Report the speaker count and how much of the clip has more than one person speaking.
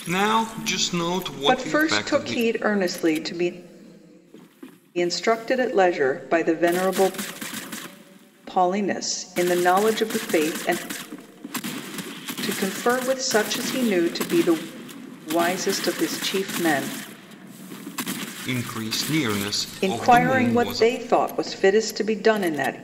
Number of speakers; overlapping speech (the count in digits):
2, about 9%